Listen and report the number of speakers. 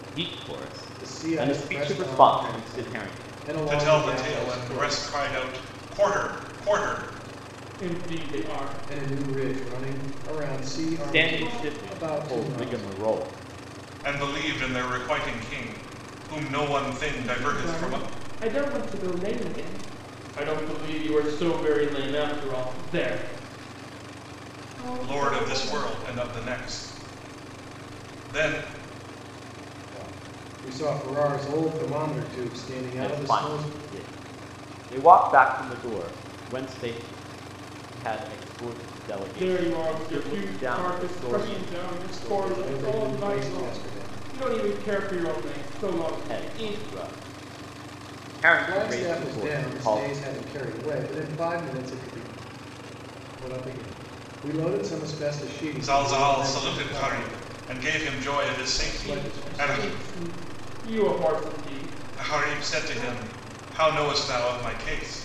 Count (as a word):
four